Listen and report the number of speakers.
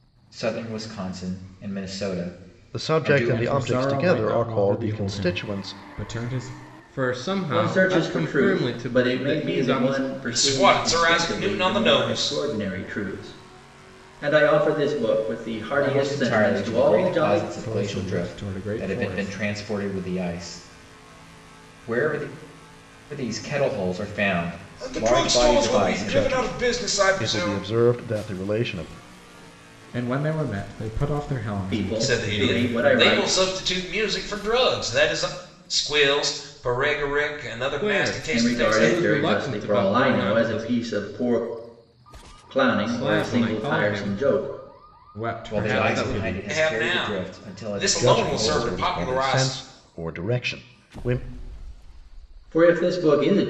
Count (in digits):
6